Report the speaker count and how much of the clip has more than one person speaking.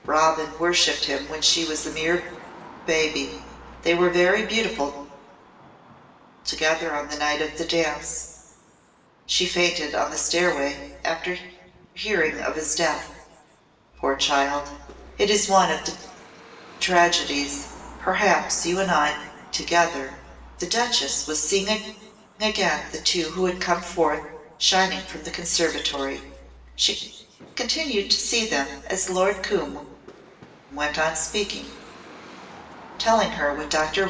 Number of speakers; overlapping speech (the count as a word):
one, no overlap